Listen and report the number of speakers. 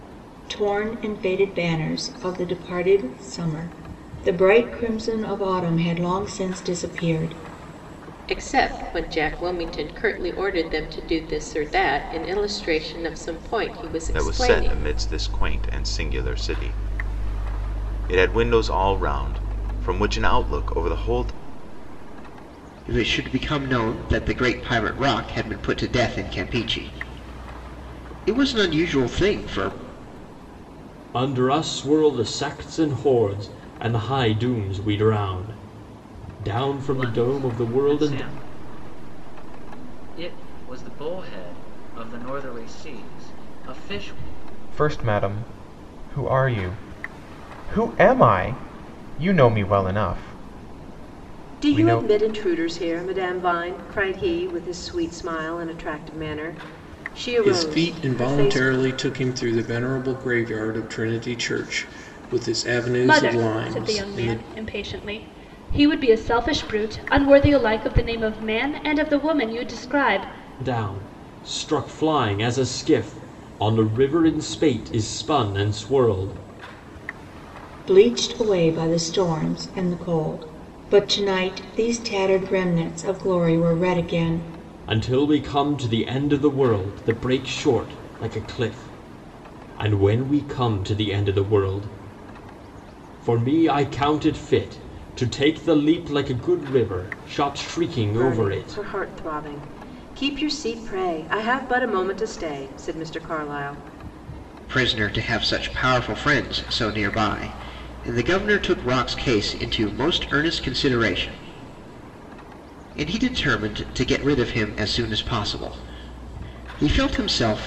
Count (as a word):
ten